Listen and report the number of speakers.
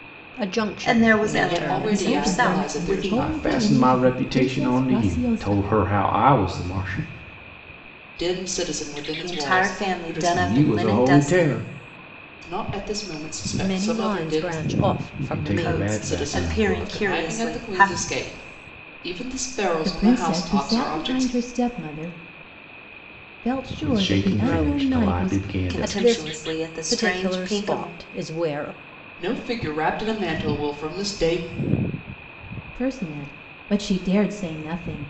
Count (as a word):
five